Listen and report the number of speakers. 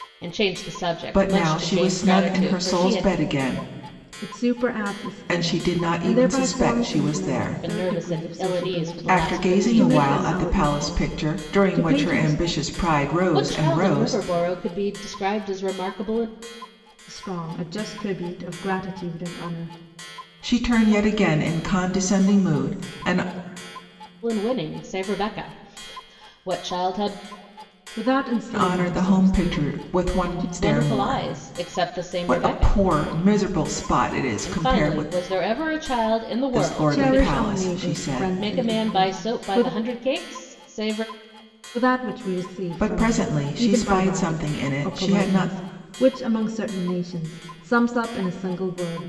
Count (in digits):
3